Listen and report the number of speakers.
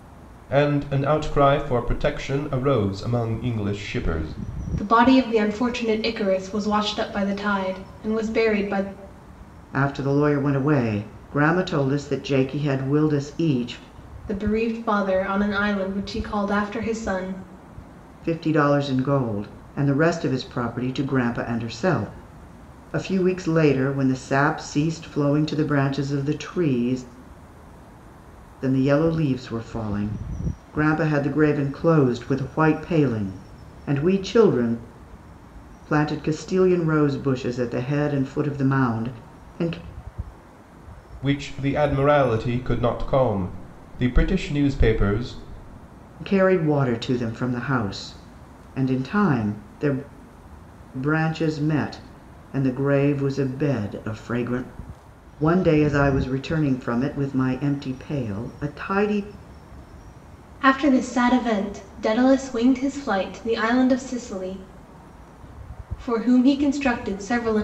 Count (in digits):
3